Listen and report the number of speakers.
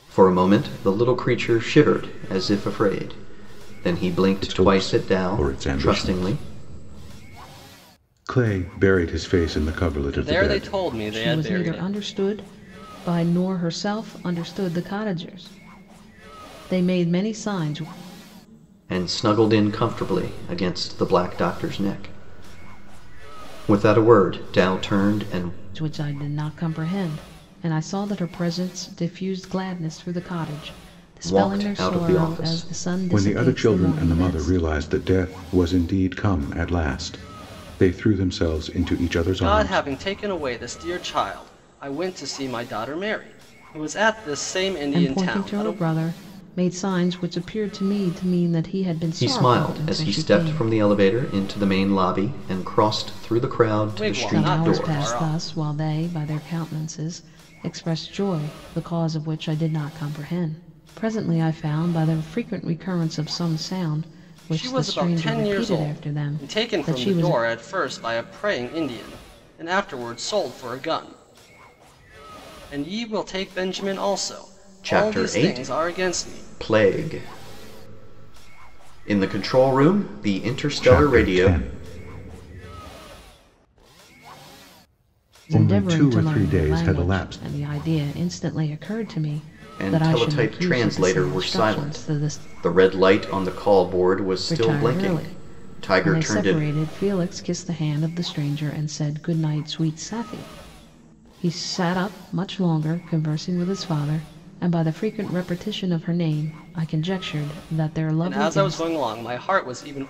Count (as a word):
four